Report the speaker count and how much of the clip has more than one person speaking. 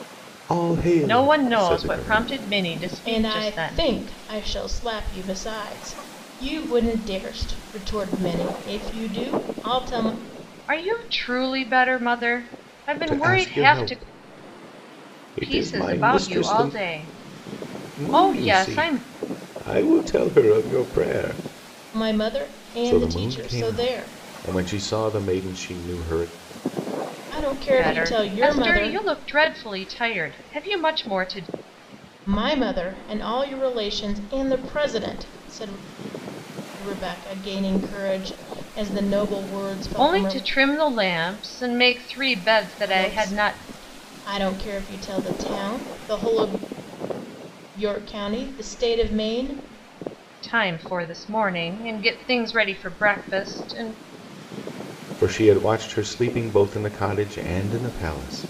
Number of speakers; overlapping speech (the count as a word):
three, about 16%